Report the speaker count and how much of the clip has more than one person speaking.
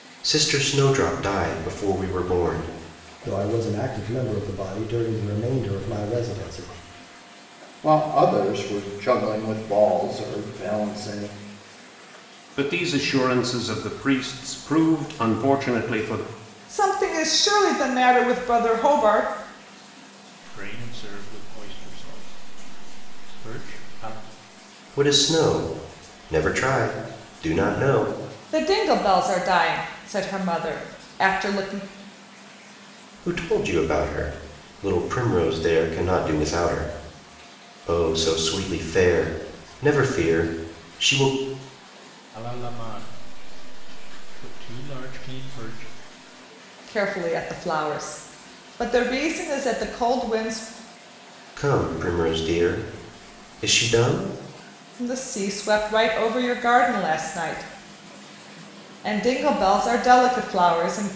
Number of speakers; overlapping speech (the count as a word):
six, no overlap